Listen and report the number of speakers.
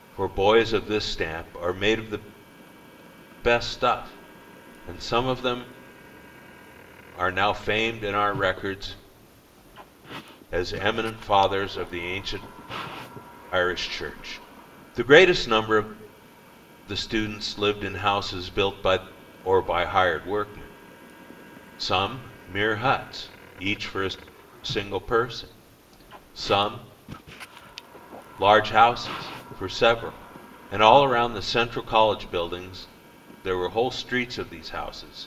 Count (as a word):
one